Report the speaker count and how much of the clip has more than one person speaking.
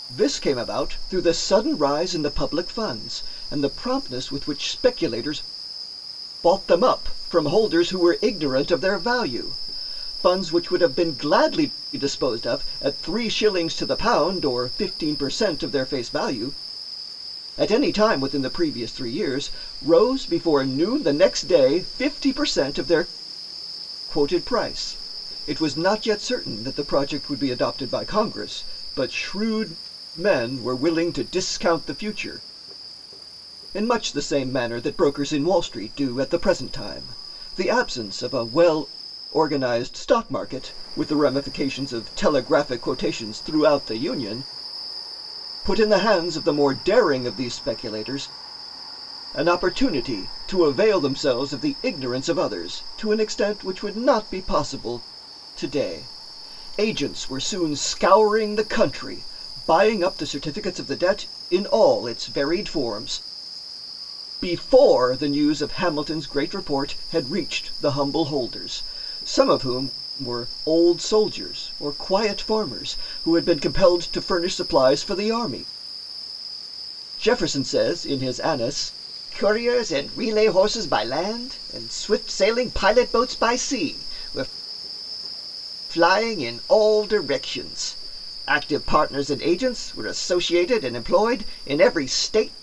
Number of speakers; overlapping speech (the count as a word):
one, no overlap